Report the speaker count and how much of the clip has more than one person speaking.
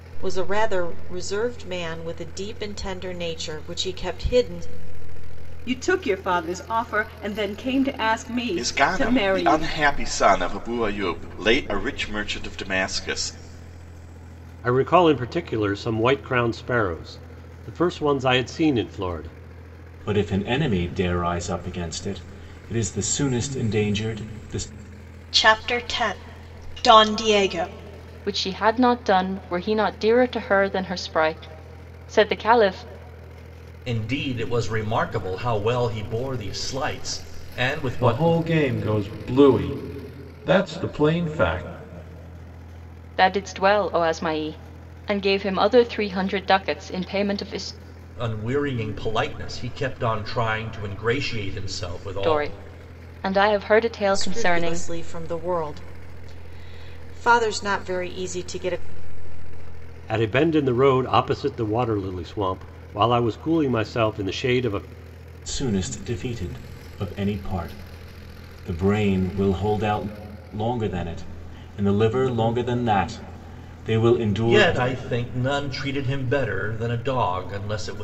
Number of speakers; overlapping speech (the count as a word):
nine, about 4%